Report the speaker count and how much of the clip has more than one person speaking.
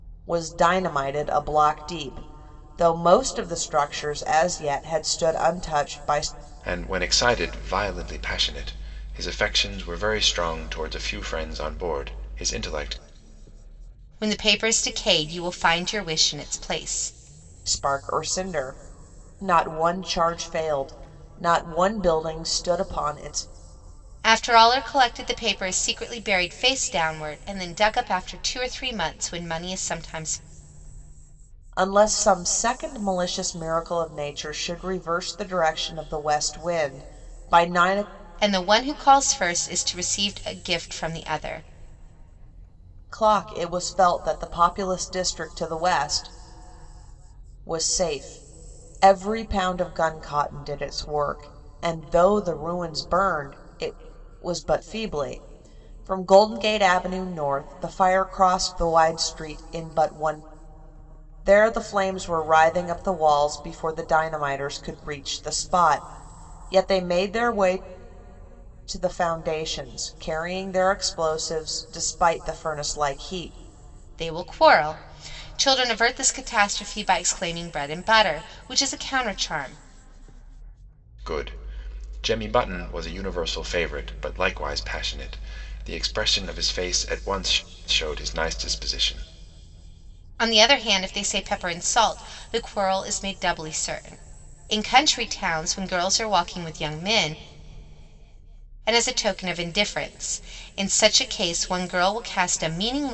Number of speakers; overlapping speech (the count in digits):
3, no overlap